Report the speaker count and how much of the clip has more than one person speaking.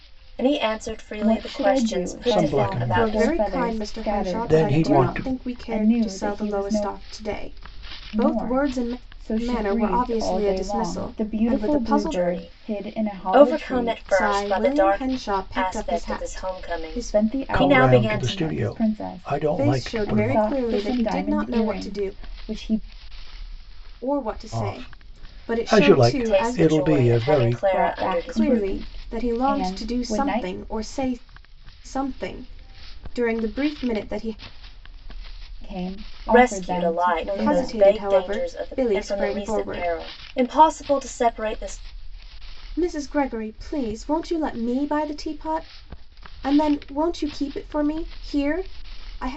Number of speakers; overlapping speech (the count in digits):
4, about 57%